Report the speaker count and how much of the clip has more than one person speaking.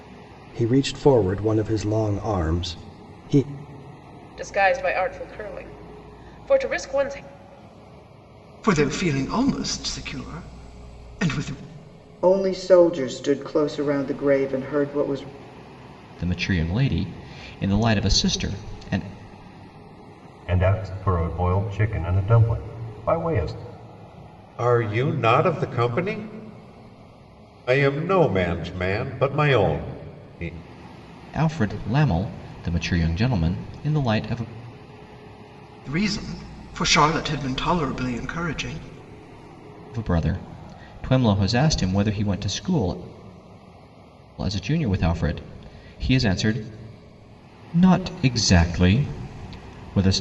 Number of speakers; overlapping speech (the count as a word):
seven, no overlap